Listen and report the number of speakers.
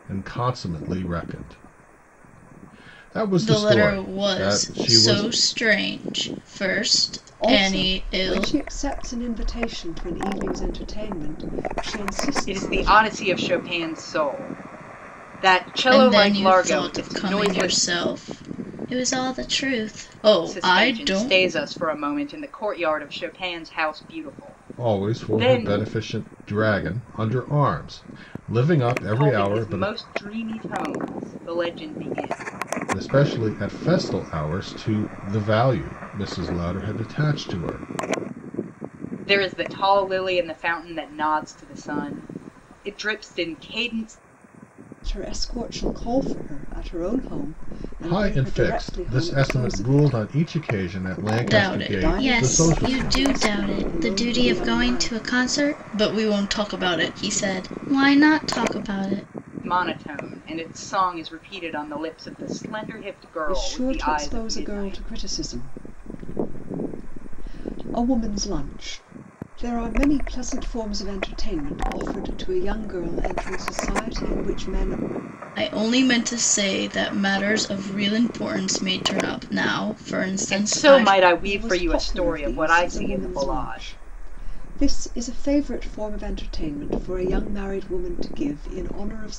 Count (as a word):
four